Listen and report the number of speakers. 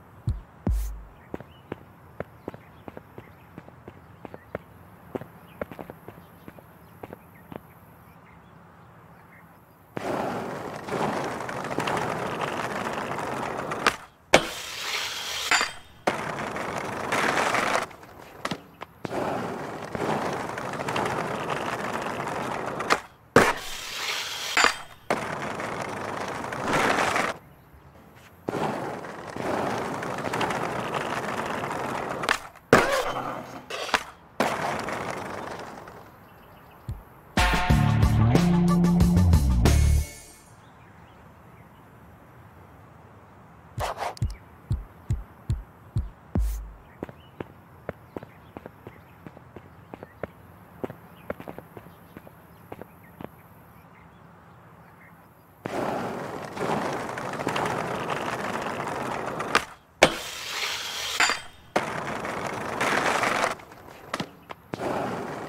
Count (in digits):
0